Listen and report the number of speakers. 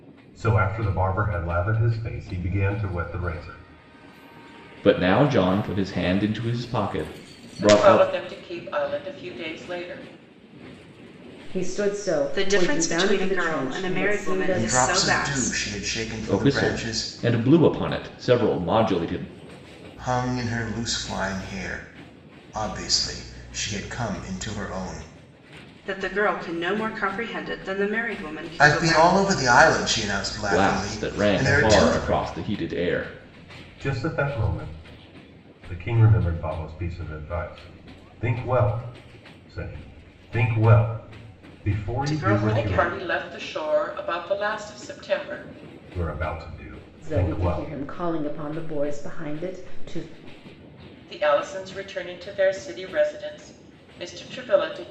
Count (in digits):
6